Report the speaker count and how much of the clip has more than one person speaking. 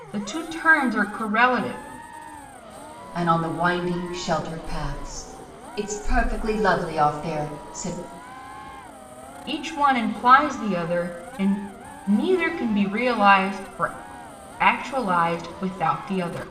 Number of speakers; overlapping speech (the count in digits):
2, no overlap